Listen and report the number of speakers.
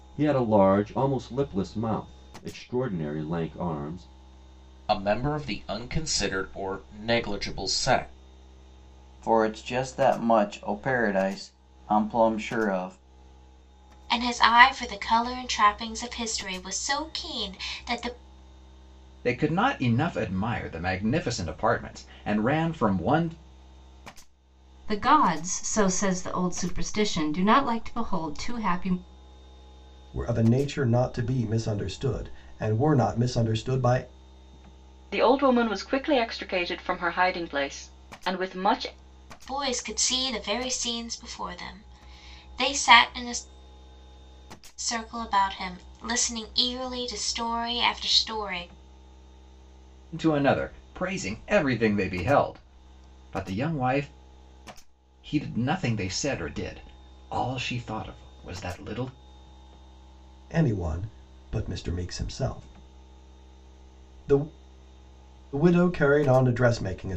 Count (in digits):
8